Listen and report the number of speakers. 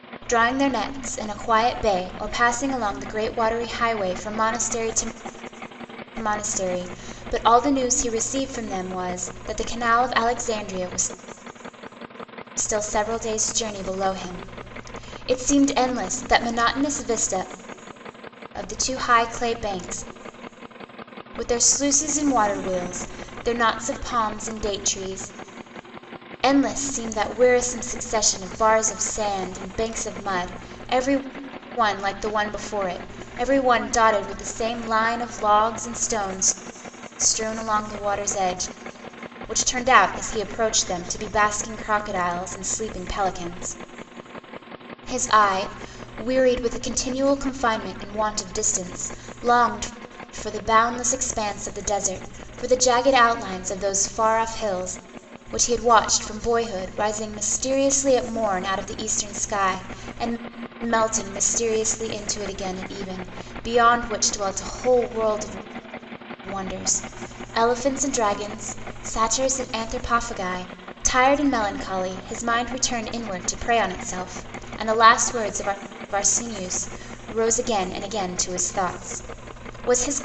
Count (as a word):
one